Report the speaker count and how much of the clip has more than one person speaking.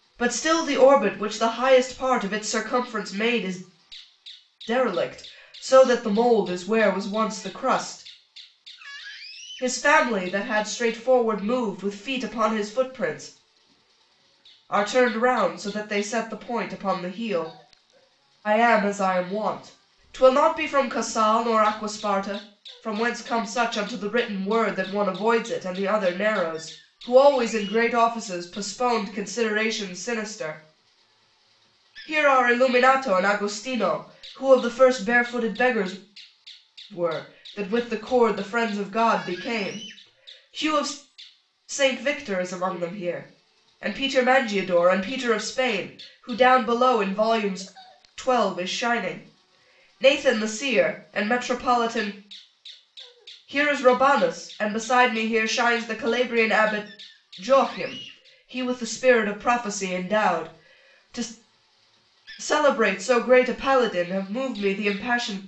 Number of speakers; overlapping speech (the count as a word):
one, no overlap